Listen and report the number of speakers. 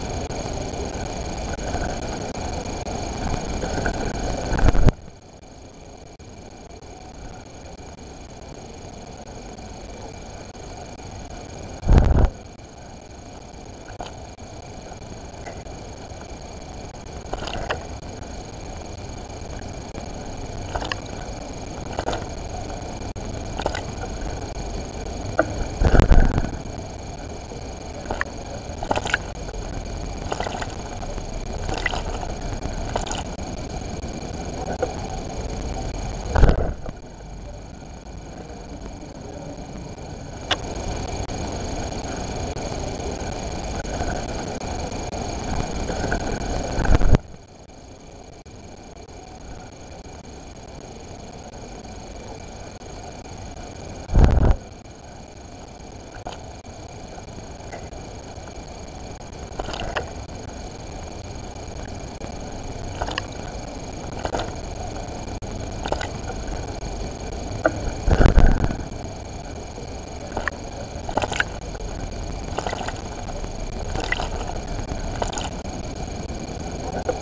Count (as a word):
zero